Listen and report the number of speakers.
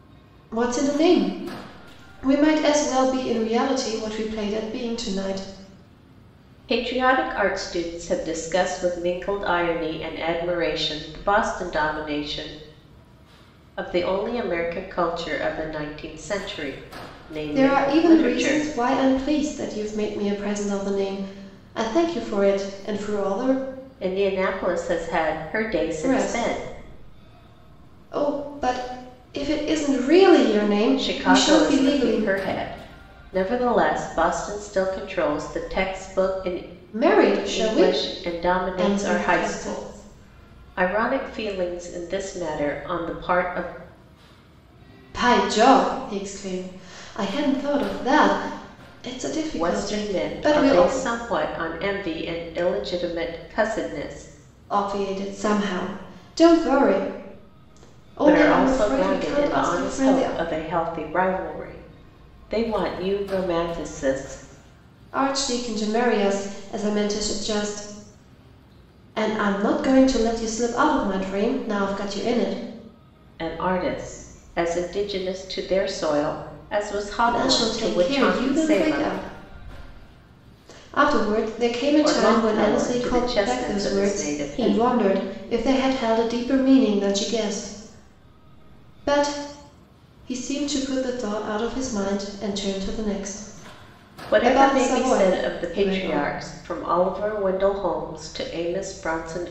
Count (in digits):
2